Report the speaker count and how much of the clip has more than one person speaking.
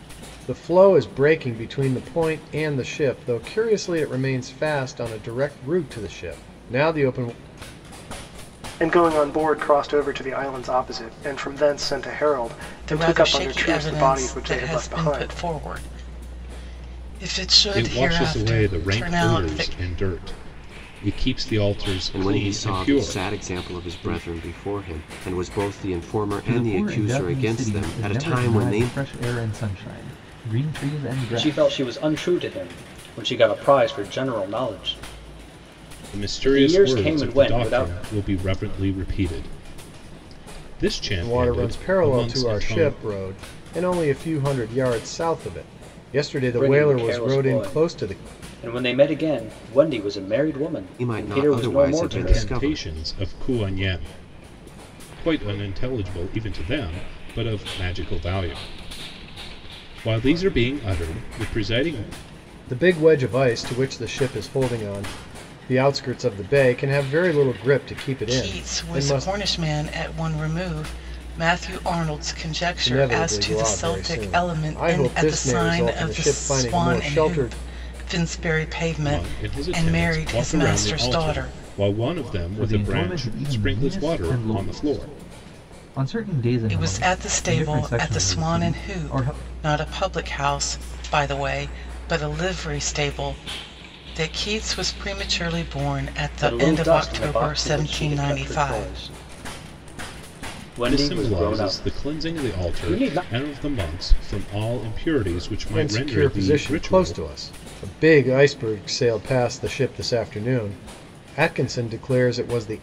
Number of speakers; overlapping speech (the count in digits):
7, about 33%